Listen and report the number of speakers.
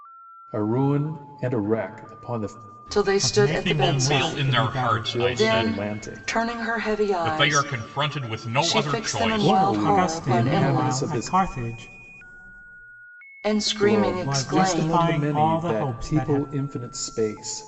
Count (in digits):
4